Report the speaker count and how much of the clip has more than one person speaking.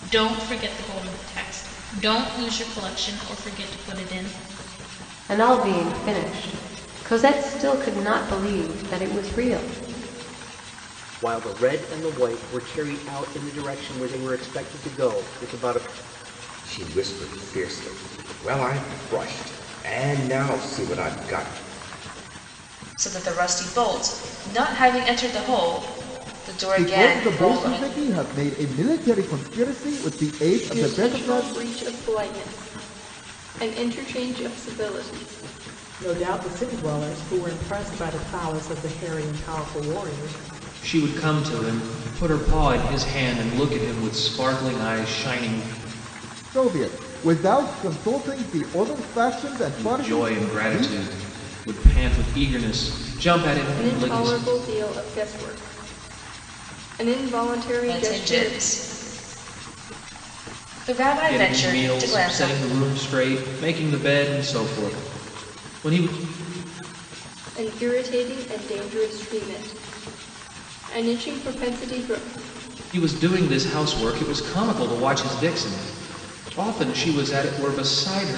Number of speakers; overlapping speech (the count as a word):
nine, about 7%